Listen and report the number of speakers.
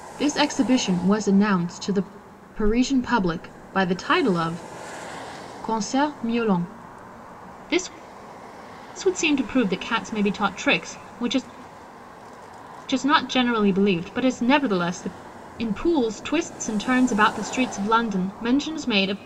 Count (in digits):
1